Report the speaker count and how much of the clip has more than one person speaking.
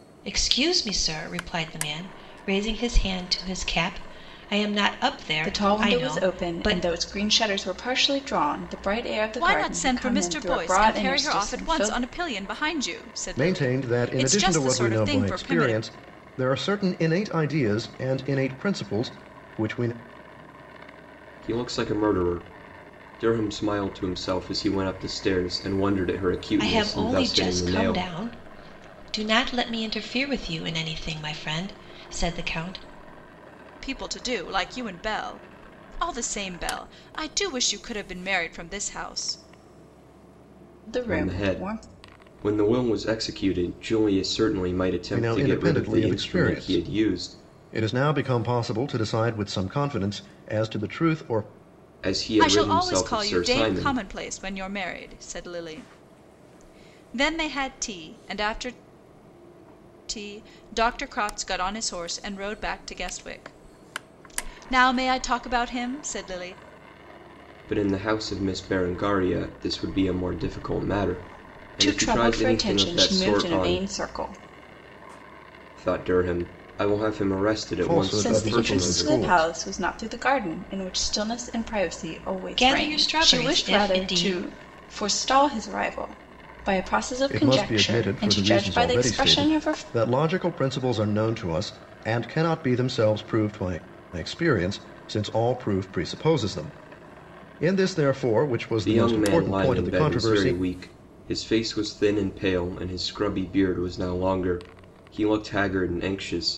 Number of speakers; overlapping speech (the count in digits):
5, about 22%